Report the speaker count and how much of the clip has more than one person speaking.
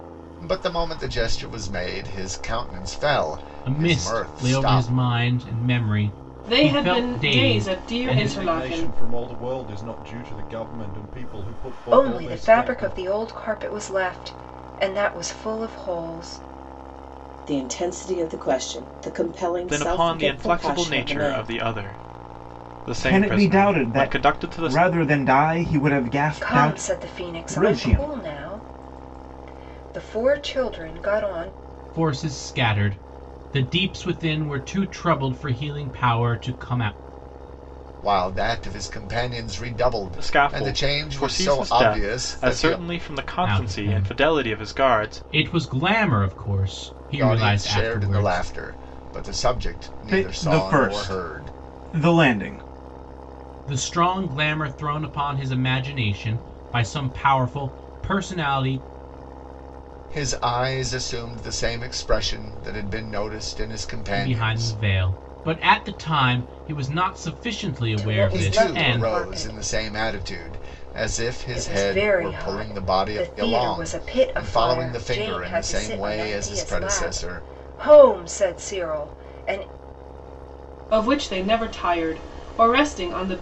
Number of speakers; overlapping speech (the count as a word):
eight, about 31%